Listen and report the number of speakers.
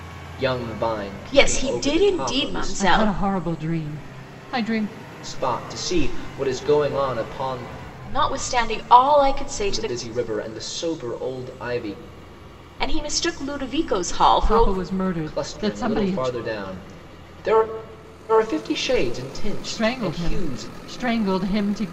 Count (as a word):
three